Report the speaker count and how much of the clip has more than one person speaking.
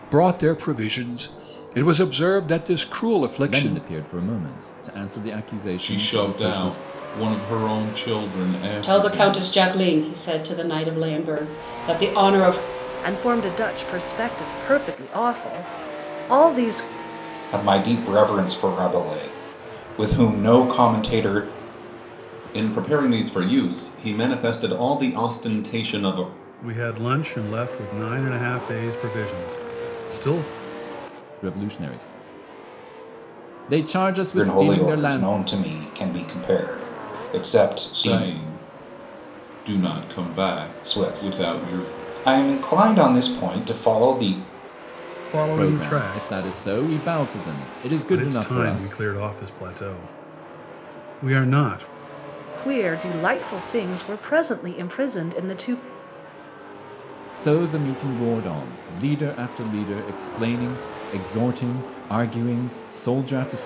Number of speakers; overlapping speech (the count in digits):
8, about 10%